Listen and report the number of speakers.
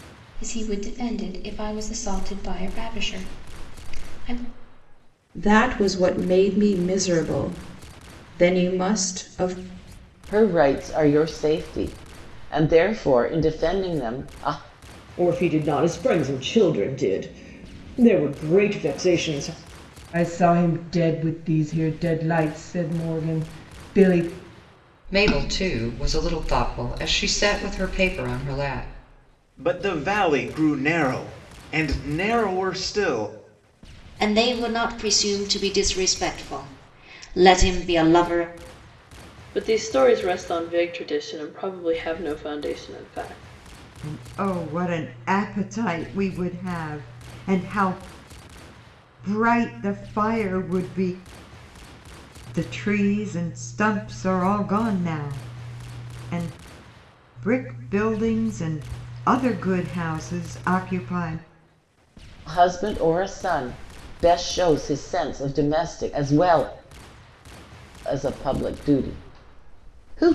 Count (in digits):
10